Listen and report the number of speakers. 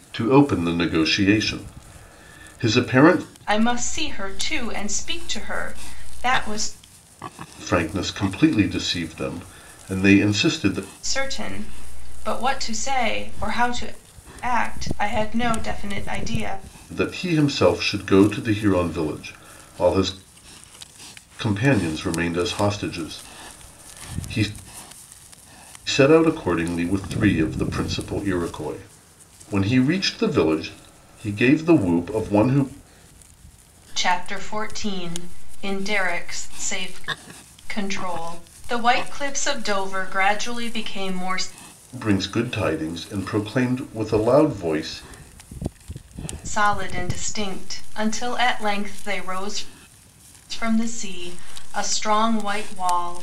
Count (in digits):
2